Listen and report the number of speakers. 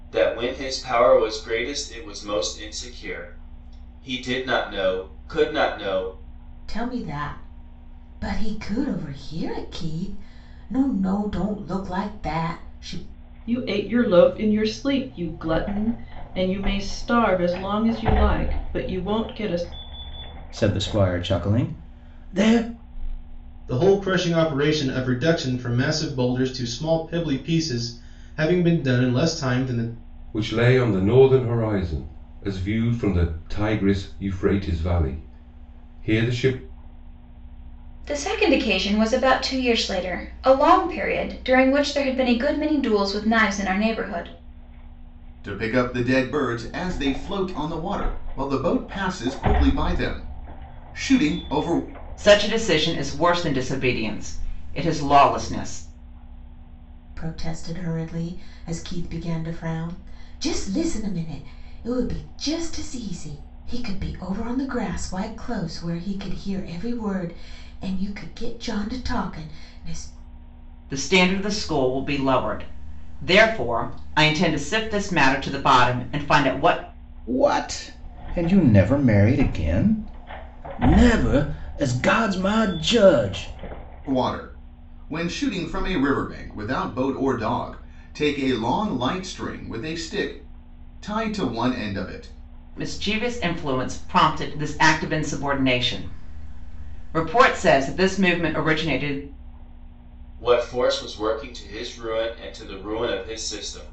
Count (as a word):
nine